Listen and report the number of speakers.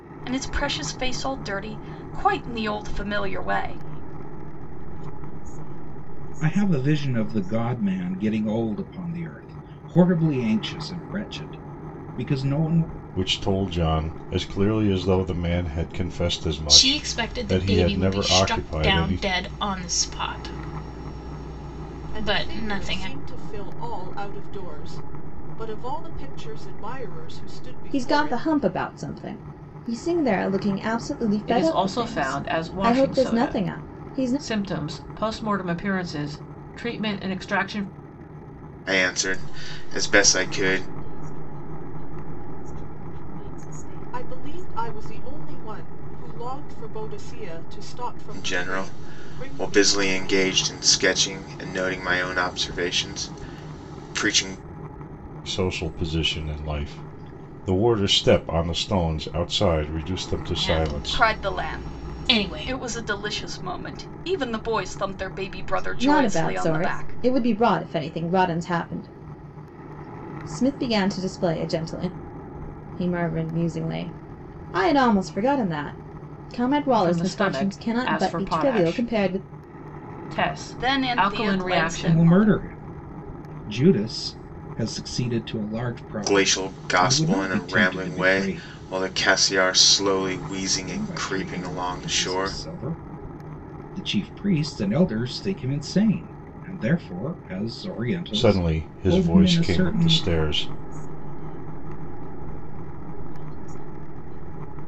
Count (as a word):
nine